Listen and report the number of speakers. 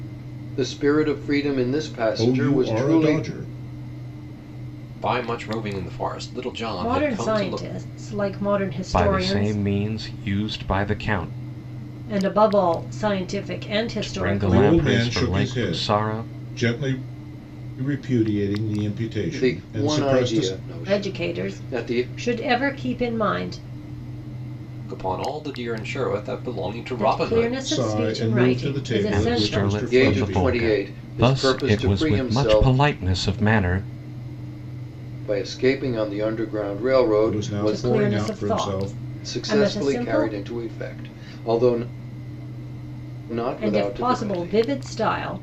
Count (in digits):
5